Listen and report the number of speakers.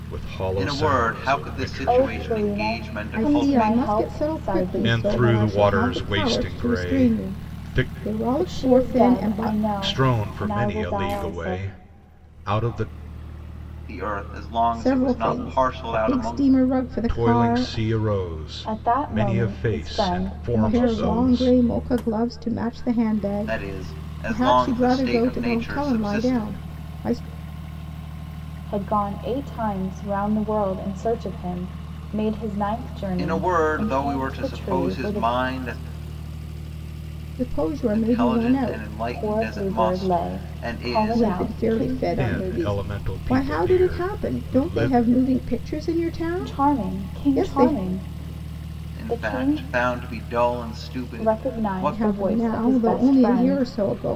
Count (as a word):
four